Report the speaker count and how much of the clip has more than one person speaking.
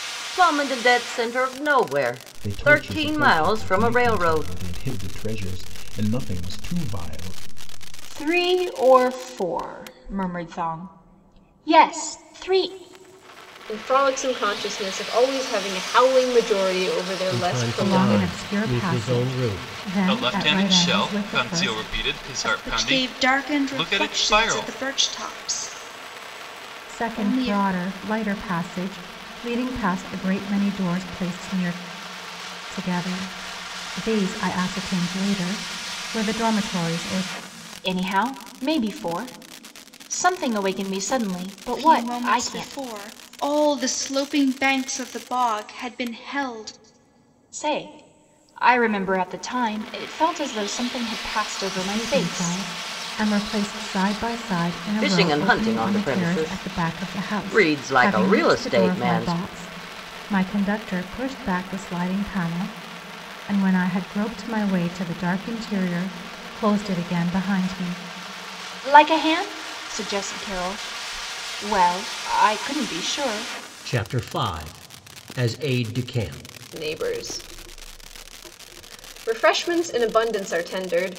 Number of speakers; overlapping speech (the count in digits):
8, about 20%